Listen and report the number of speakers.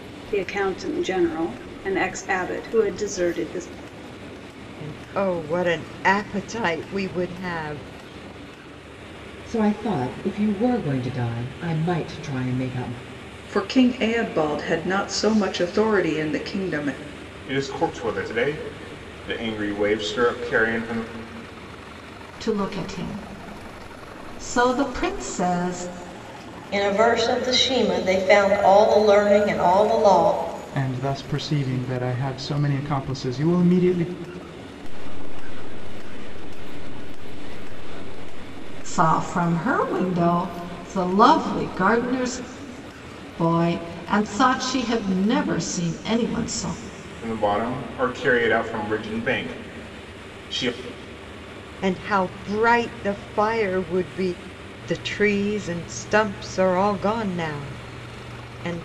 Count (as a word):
nine